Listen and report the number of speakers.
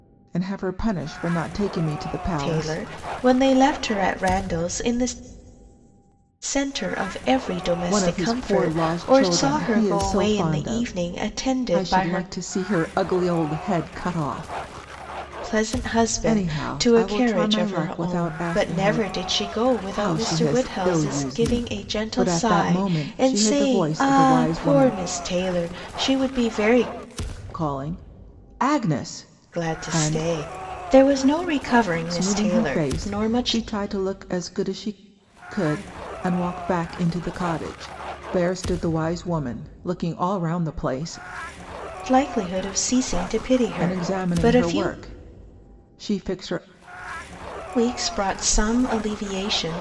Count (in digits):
2